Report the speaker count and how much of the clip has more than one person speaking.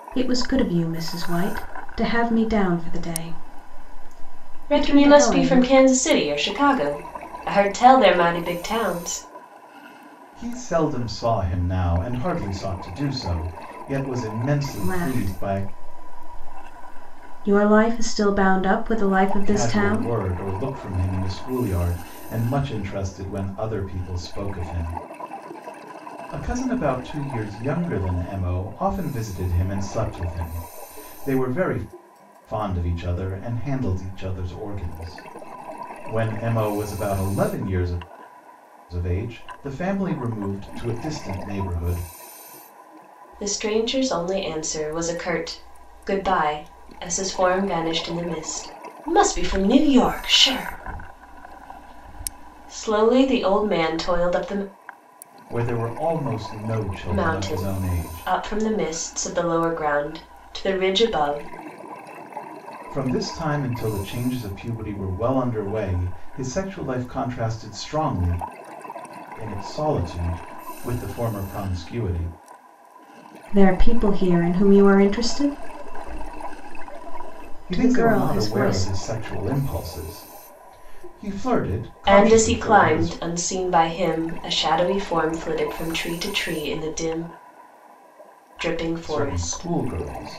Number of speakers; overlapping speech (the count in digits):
3, about 8%